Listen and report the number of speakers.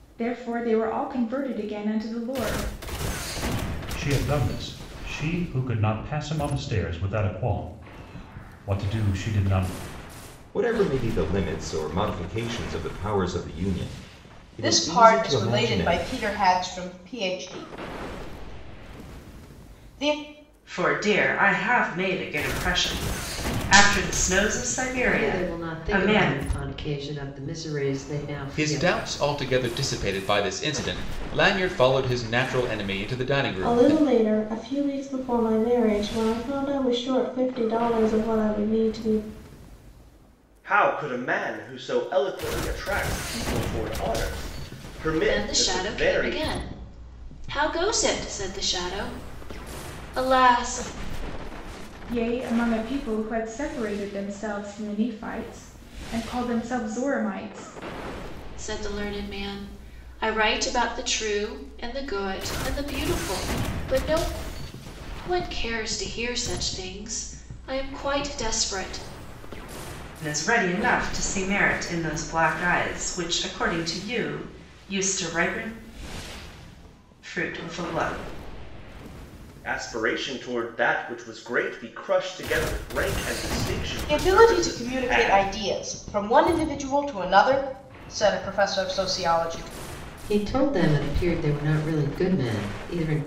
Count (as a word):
ten